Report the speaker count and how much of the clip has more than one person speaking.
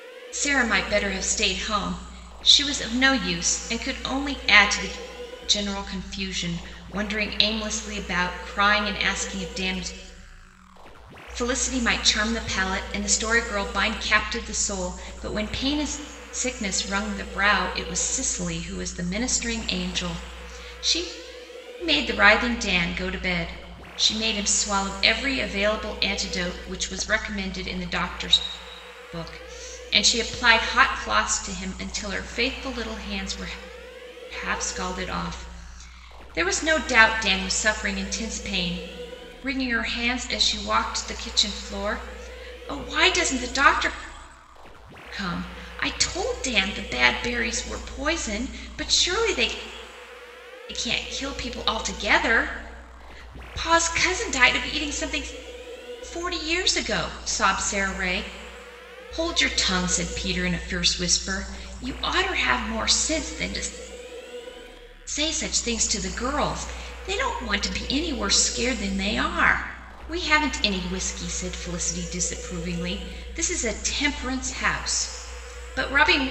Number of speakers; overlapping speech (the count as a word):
one, no overlap